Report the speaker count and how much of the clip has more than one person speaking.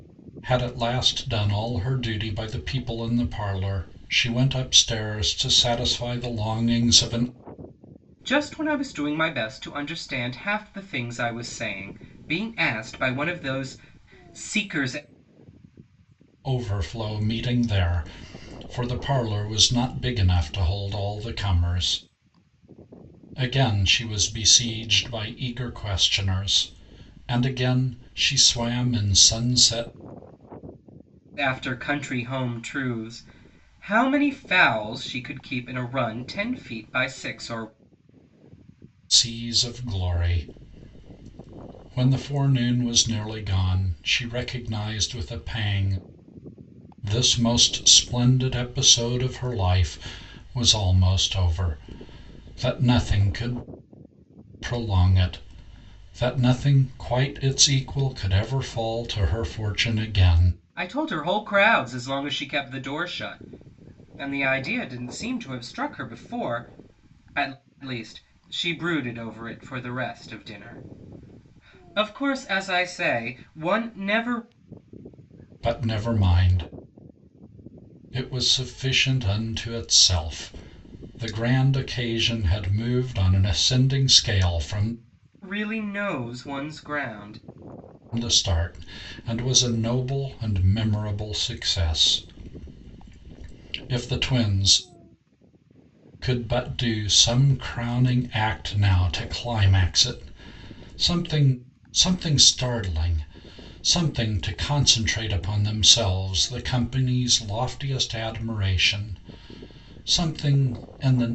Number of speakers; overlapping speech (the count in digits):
2, no overlap